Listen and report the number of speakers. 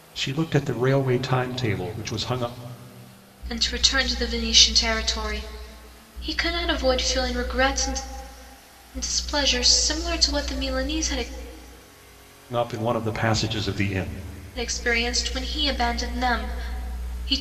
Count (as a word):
two